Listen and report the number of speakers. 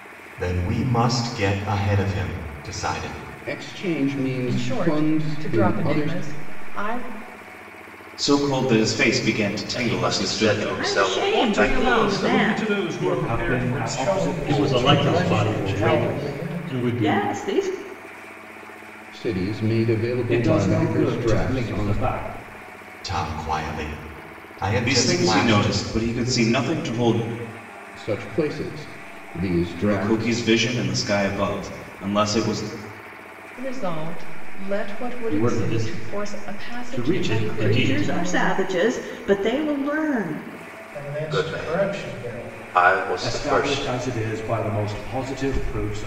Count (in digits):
10